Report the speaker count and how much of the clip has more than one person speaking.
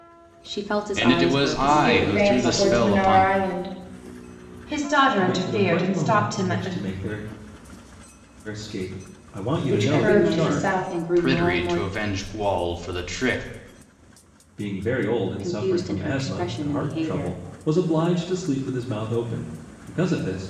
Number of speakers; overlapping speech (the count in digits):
5, about 41%